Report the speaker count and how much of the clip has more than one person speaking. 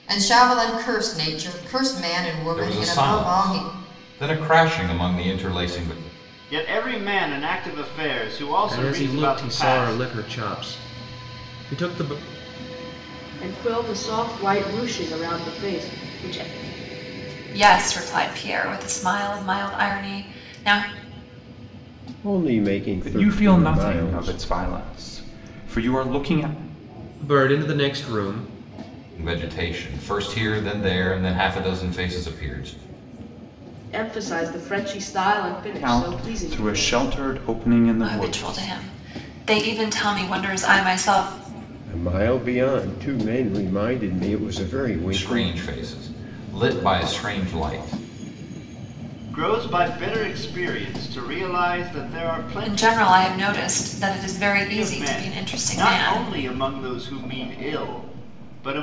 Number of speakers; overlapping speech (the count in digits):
8, about 14%